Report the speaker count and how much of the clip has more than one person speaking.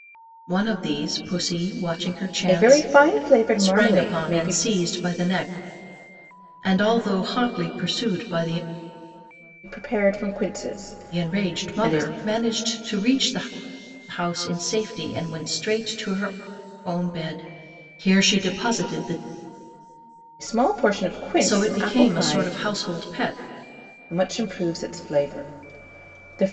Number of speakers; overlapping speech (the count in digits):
2, about 13%